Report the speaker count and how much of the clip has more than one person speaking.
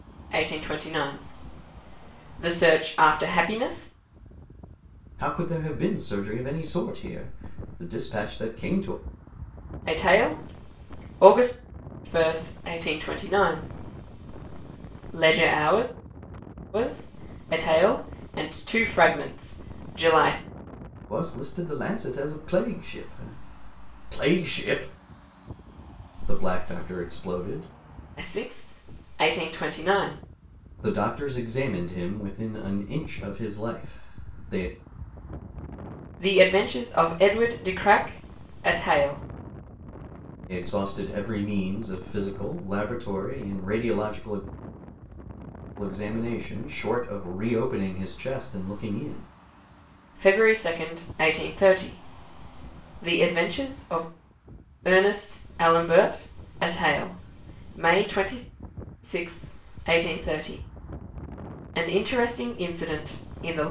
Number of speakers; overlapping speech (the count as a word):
two, no overlap